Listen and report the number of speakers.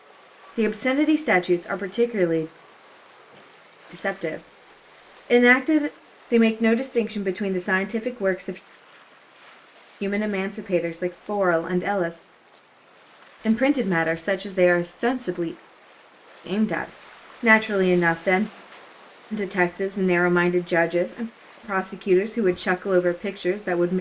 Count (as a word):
one